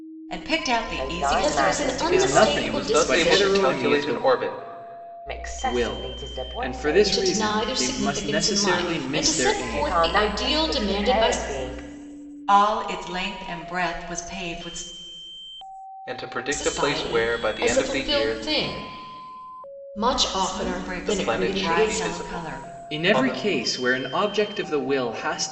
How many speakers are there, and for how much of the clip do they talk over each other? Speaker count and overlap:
5, about 54%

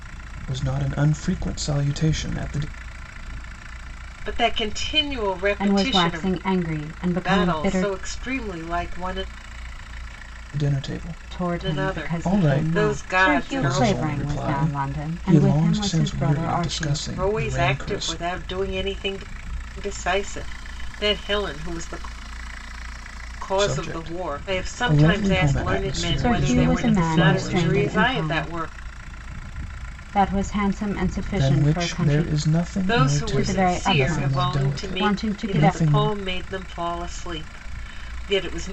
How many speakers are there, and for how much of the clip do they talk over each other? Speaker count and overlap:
3, about 46%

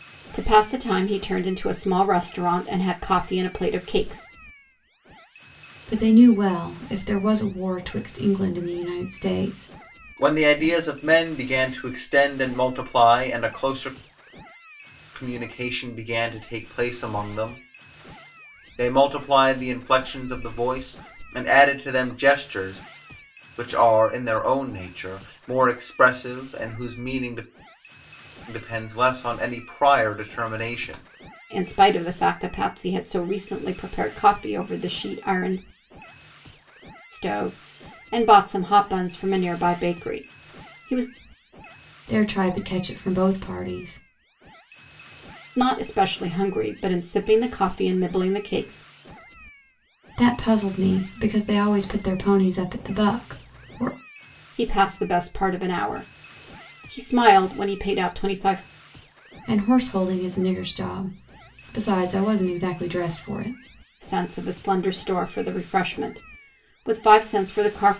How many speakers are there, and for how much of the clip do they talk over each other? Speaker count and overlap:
3, no overlap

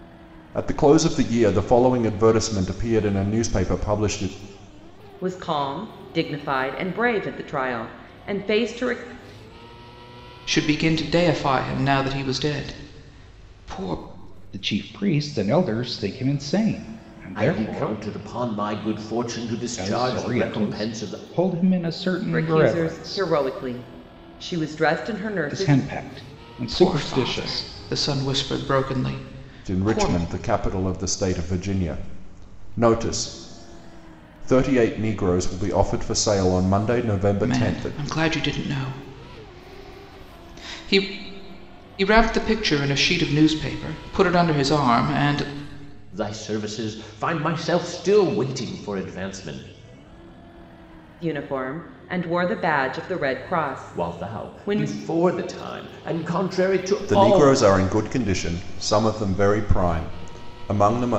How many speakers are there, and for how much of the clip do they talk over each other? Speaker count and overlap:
5, about 11%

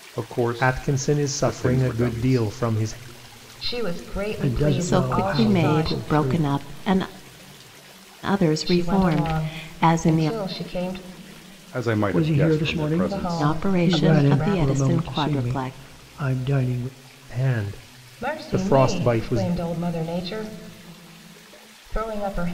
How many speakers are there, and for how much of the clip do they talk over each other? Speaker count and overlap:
5, about 48%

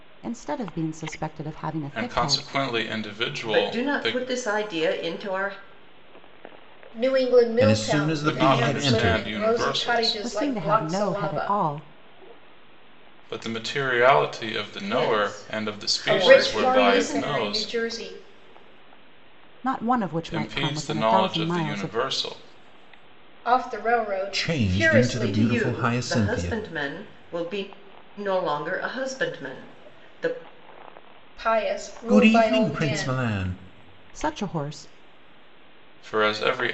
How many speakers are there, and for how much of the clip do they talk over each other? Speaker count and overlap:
5, about 37%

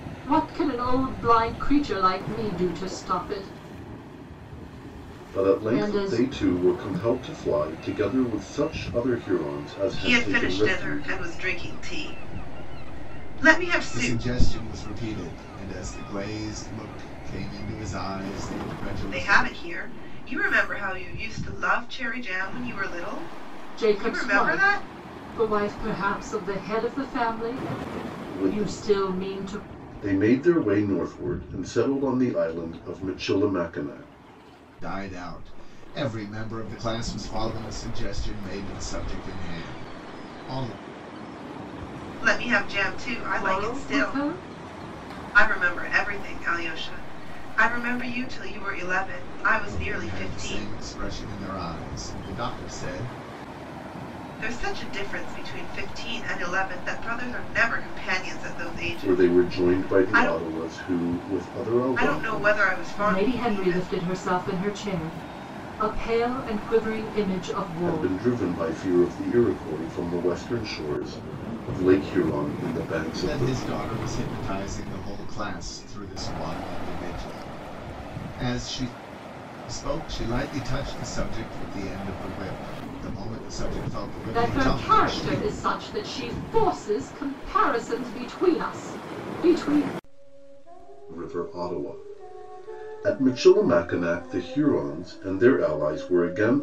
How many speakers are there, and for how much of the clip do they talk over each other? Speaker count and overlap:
4, about 14%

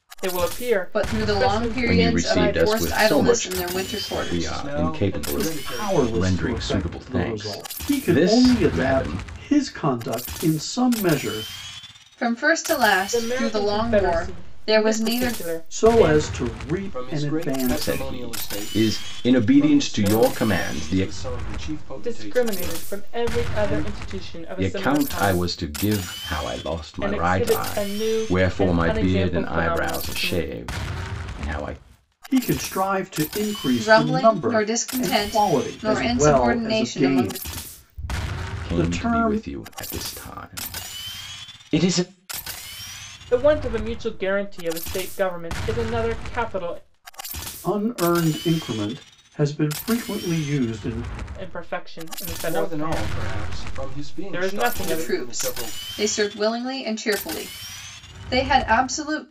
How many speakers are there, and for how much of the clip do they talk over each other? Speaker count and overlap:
5, about 49%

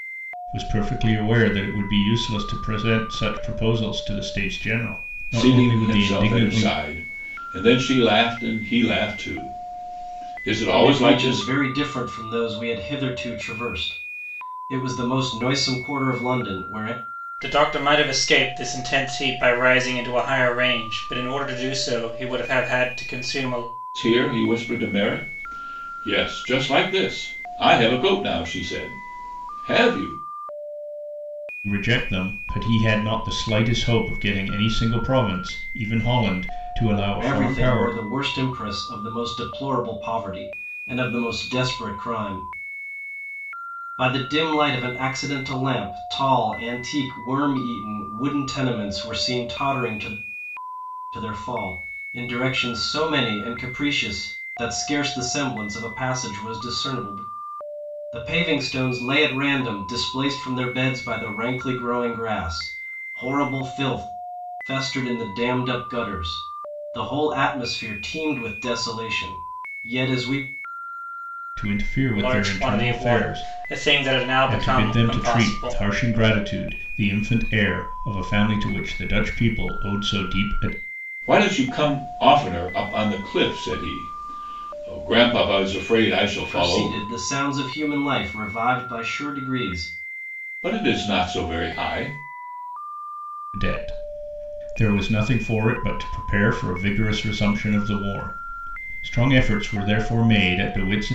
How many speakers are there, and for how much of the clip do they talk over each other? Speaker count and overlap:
4, about 6%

